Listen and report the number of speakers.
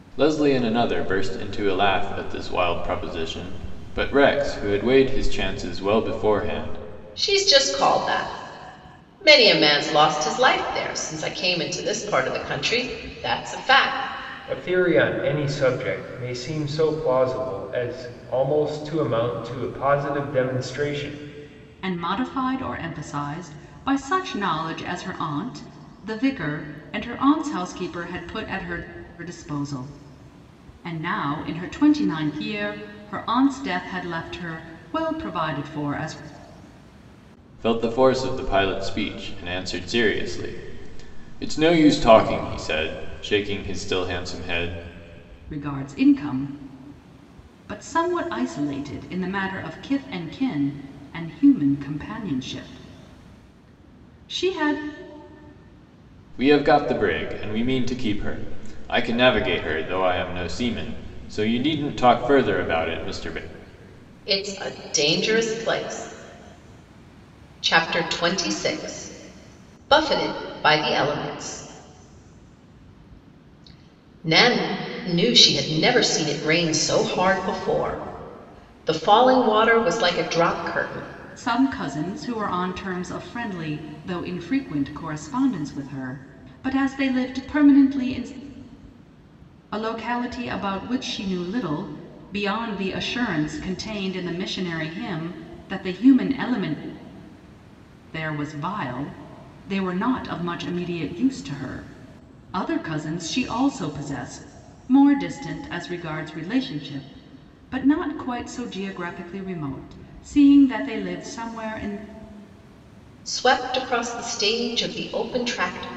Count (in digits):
4